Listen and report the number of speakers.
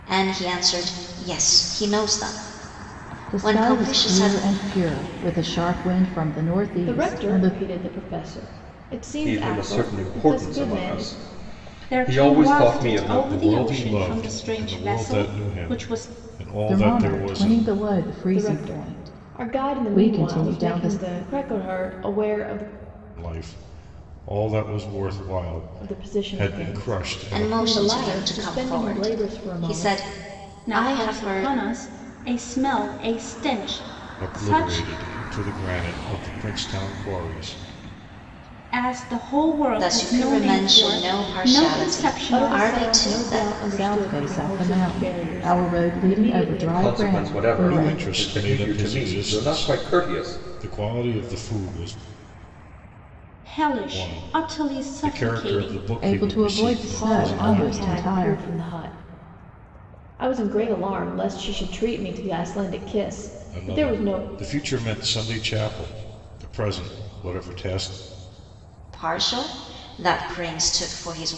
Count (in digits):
6